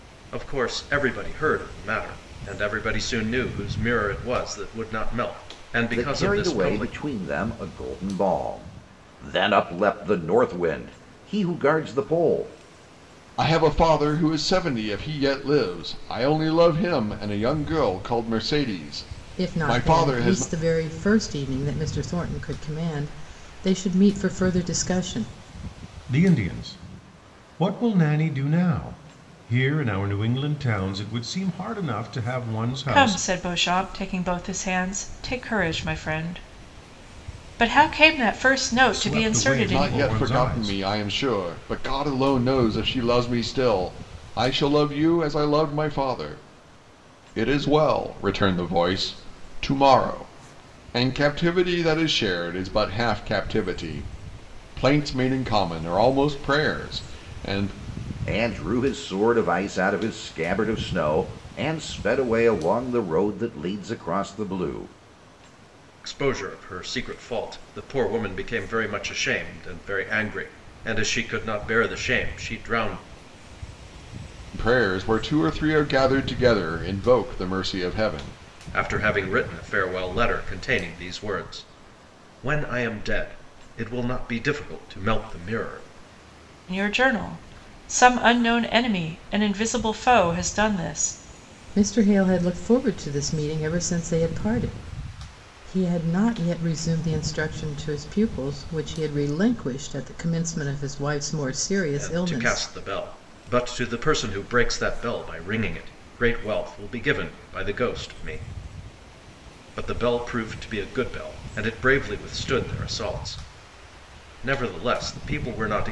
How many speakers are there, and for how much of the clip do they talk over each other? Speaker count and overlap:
6, about 5%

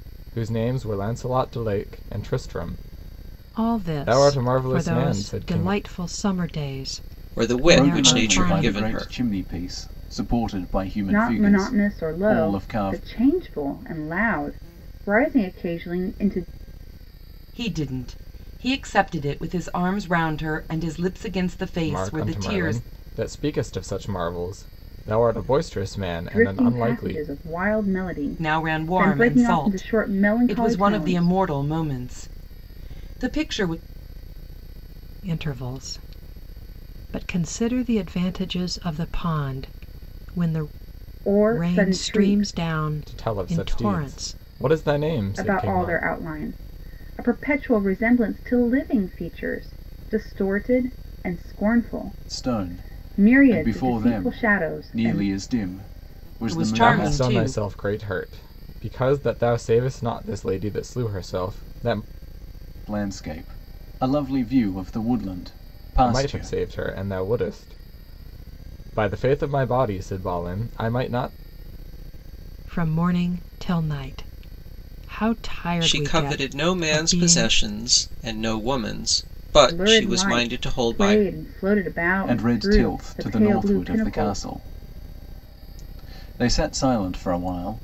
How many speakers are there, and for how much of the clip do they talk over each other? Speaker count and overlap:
6, about 28%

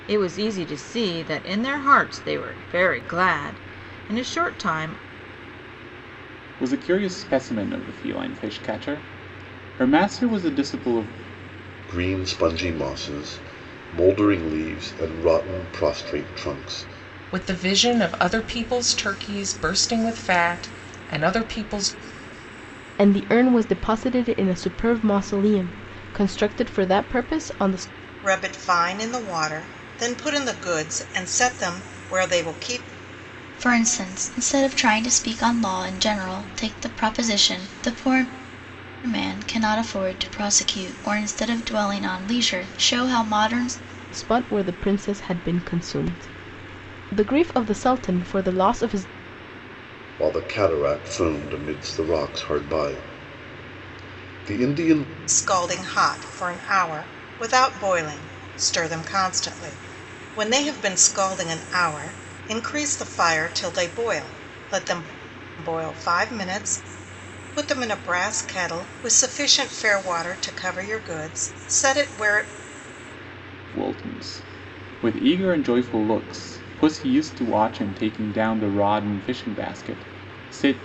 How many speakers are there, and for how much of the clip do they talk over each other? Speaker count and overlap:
7, no overlap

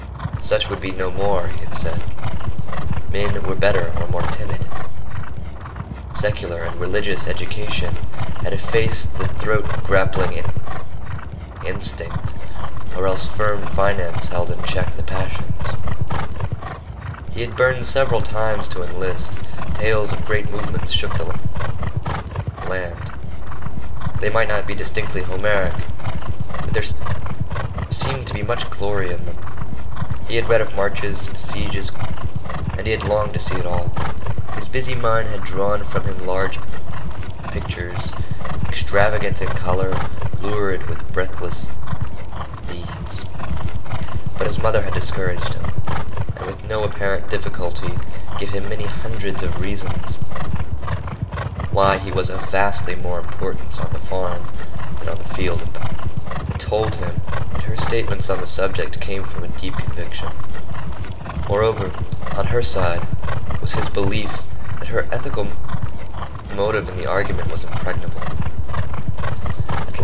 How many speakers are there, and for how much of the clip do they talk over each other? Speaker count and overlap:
1, no overlap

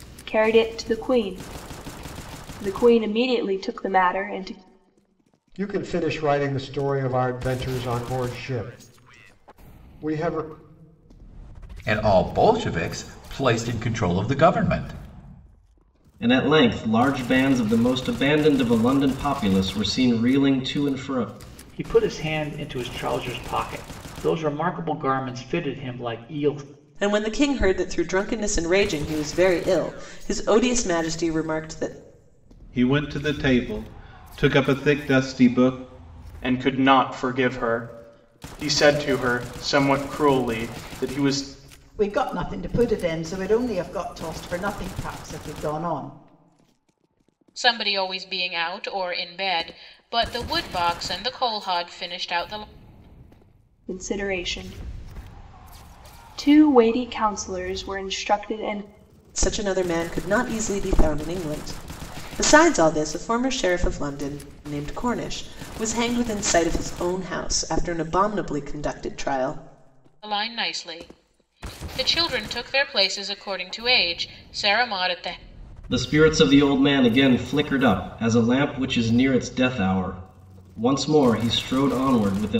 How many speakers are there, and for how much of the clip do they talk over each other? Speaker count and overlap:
10, no overlap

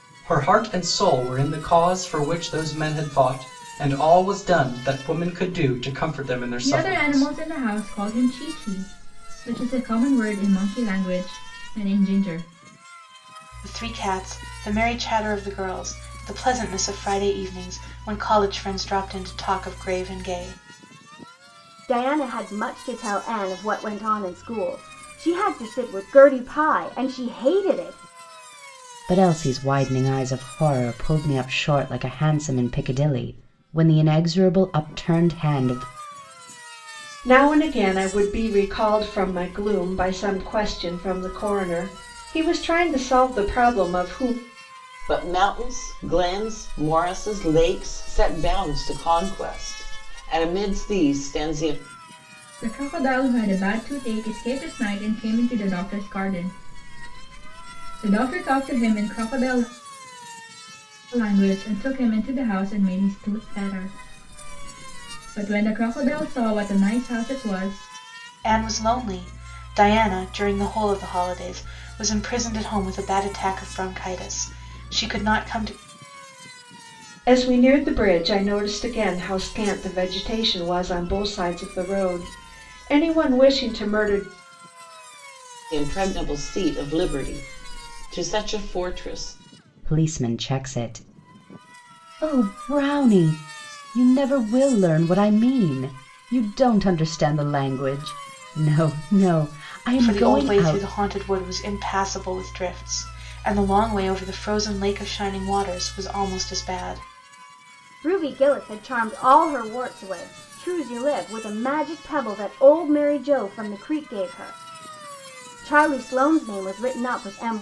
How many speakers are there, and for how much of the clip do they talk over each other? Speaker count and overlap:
7, about 1%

